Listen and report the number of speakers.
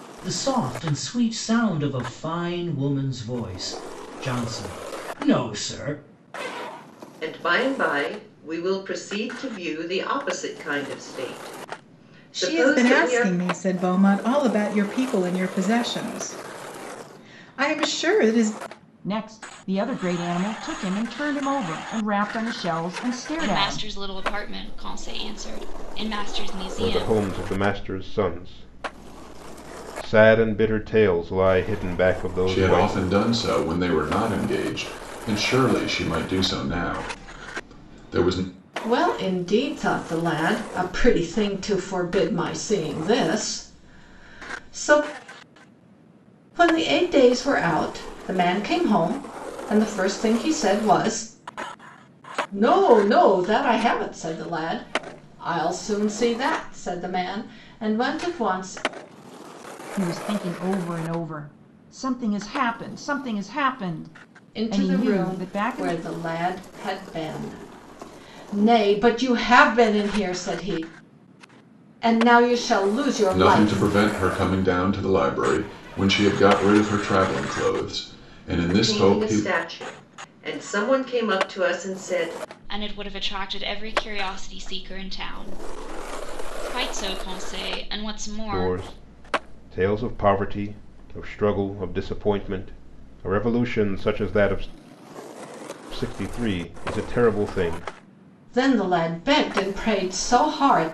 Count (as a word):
eight